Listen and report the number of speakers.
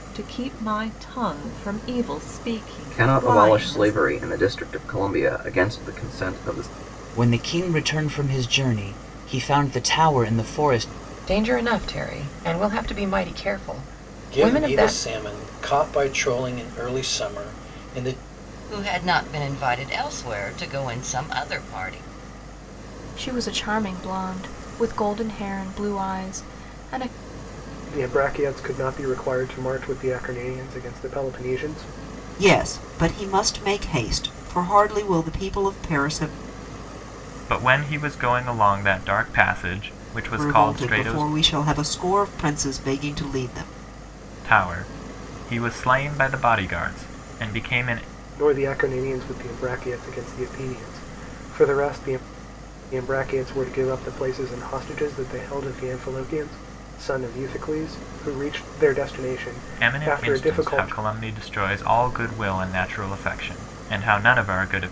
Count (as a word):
ten